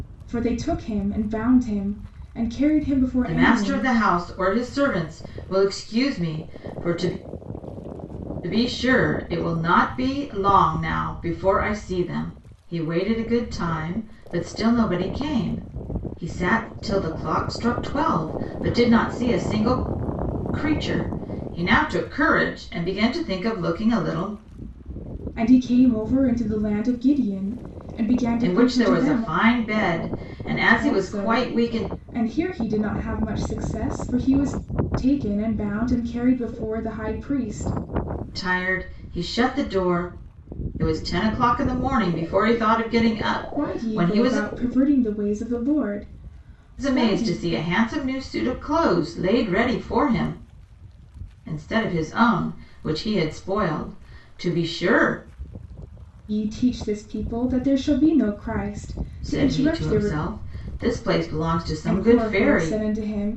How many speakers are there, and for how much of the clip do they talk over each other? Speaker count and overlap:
two, about 10%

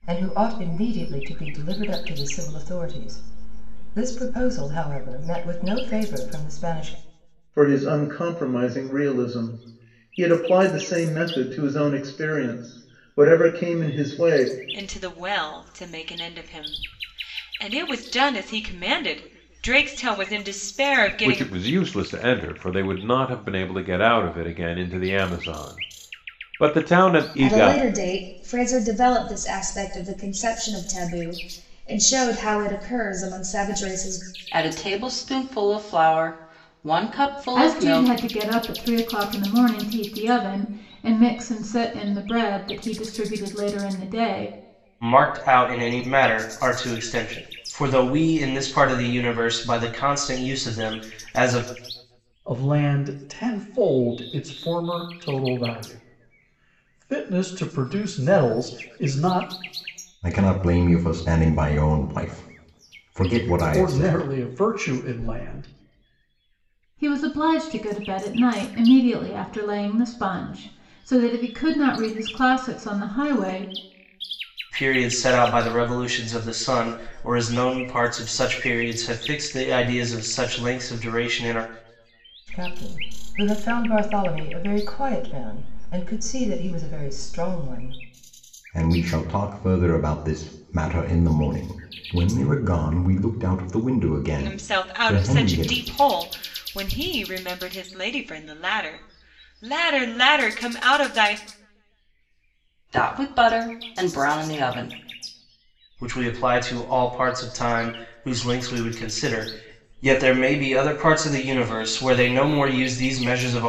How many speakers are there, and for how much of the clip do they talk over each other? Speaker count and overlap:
ten, about 3%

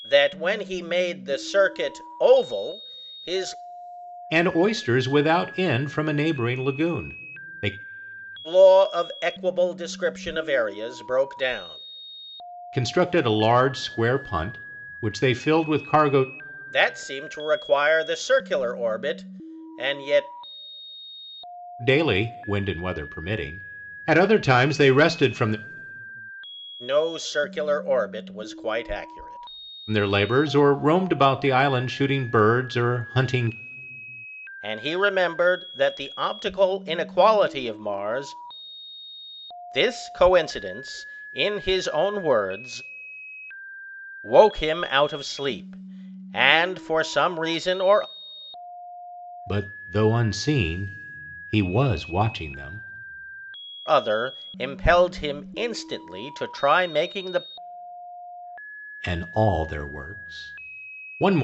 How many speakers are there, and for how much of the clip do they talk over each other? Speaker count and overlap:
two, no overlap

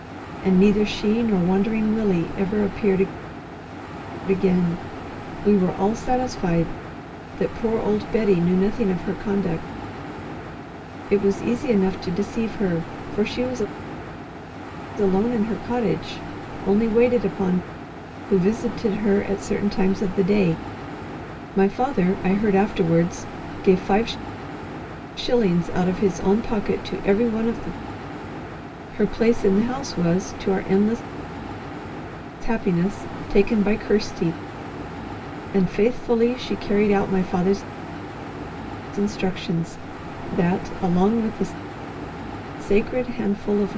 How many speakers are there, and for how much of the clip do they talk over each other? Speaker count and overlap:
one, no overlap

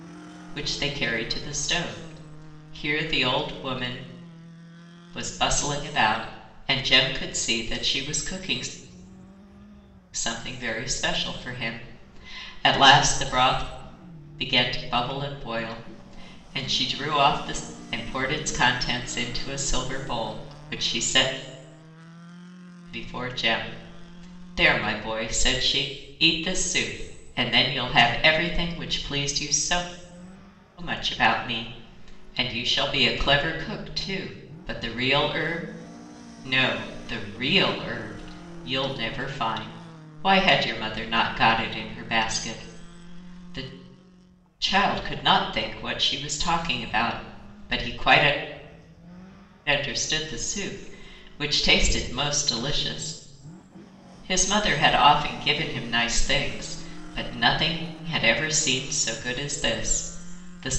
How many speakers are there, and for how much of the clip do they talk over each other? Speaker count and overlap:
one, no overlap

